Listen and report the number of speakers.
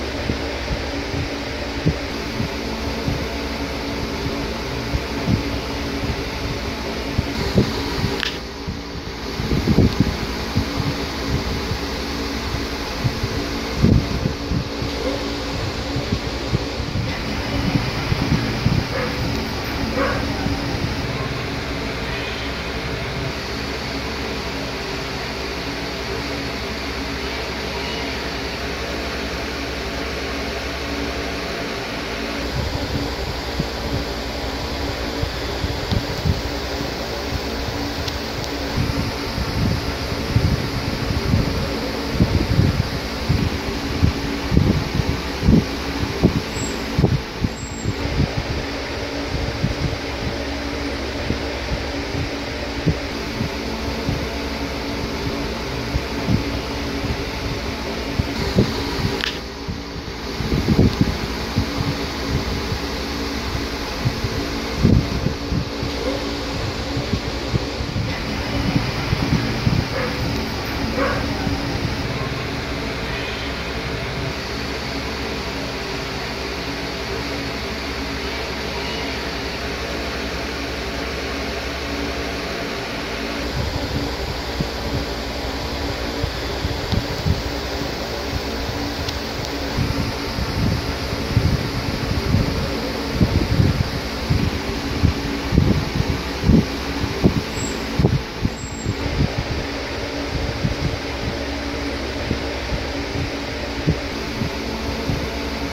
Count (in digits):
0